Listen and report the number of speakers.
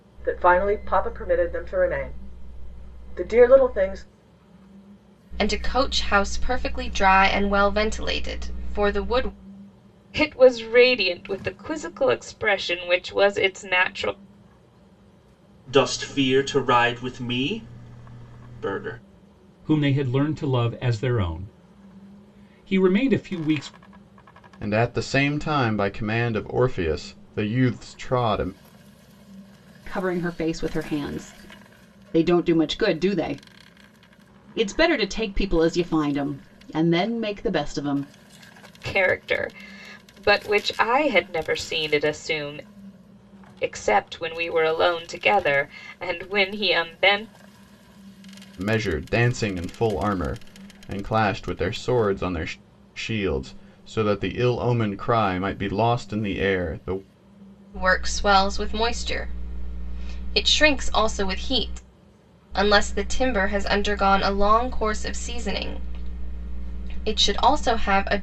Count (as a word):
seven